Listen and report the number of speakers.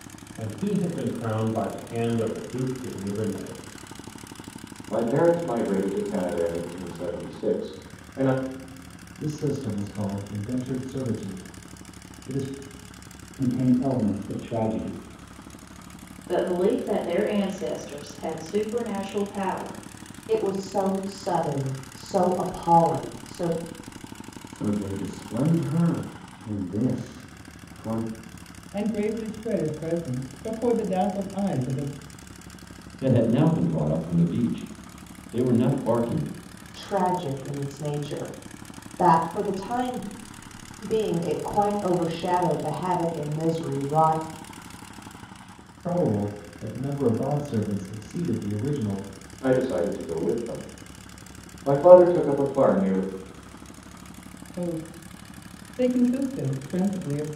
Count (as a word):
nine